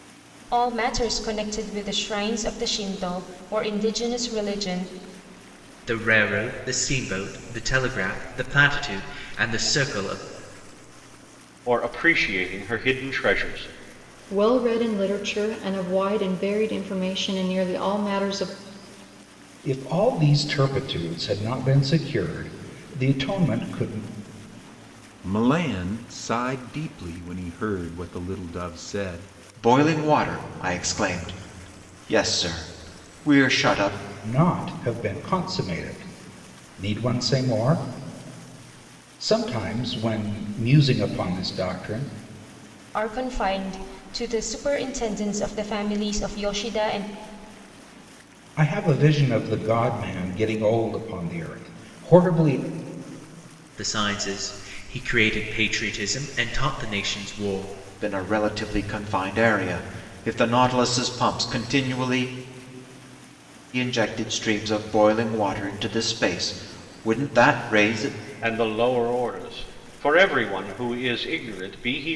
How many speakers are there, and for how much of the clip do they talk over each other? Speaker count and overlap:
7, no overlap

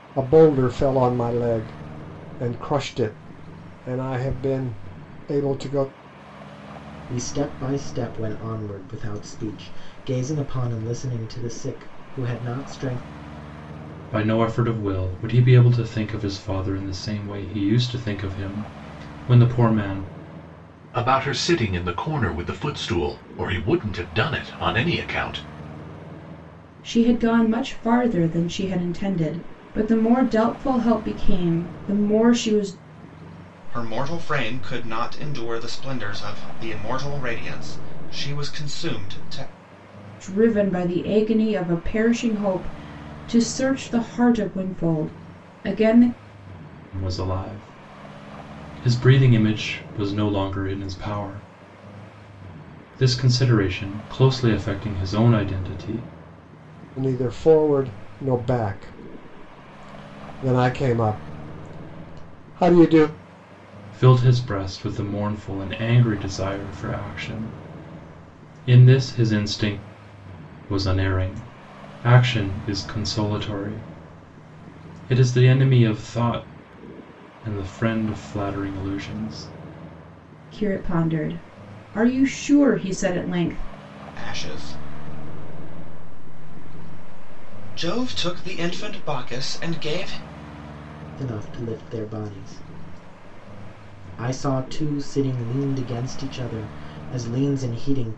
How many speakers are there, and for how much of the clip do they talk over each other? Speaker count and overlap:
6, no overlap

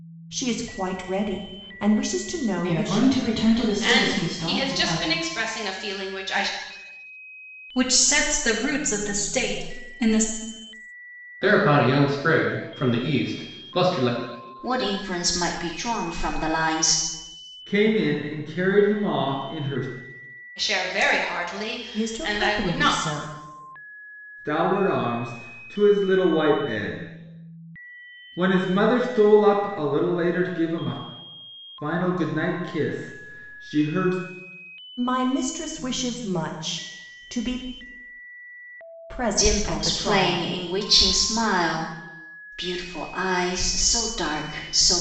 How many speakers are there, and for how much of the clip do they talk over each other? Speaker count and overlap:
7, about 9%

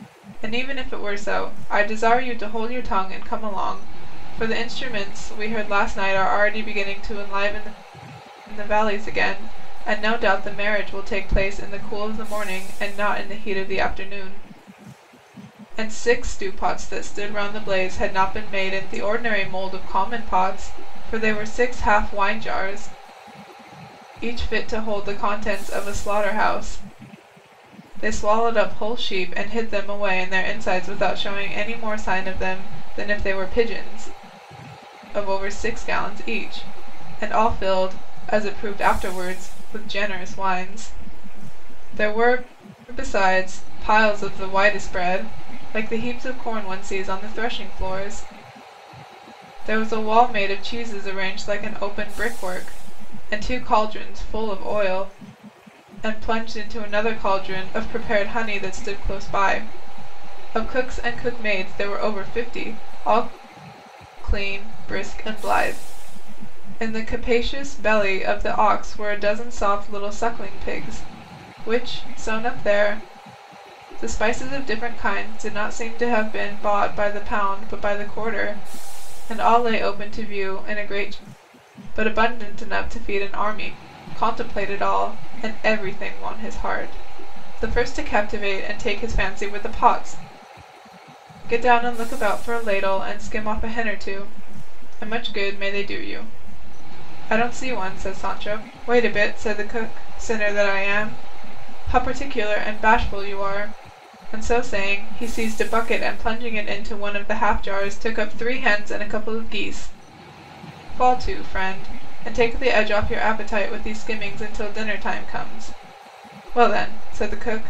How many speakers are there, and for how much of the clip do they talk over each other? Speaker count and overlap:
1, no overlap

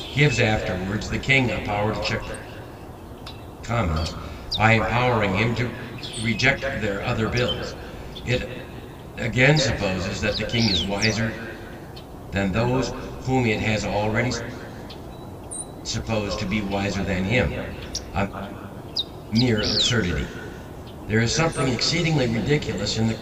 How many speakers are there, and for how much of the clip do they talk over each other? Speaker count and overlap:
1, no overlap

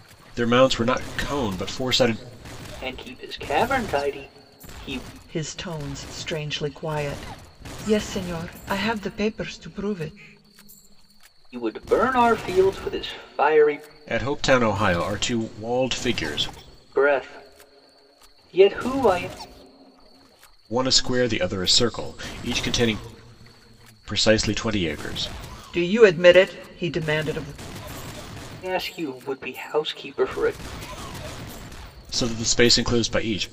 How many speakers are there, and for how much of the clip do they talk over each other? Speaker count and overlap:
3, no overlap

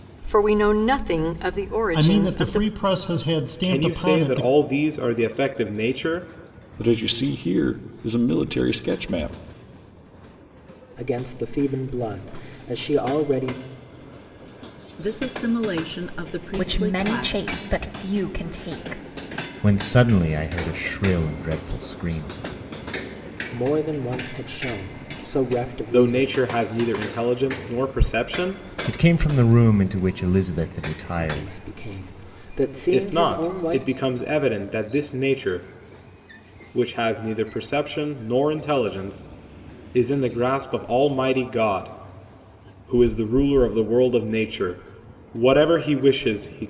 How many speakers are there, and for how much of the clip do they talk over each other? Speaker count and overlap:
8, about 10%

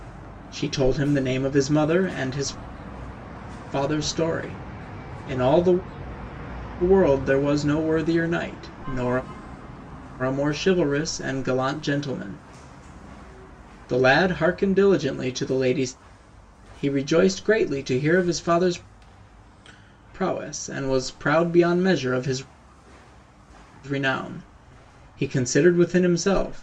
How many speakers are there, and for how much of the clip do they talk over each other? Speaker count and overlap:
1, no overlap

